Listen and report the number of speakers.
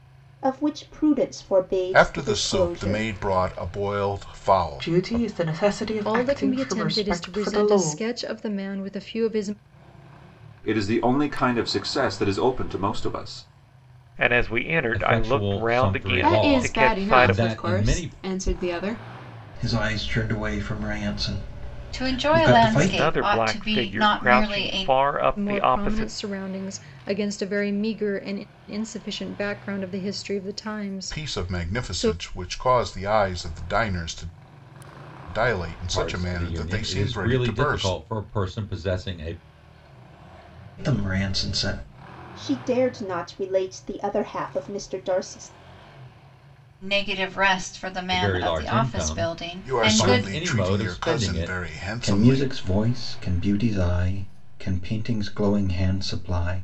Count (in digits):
10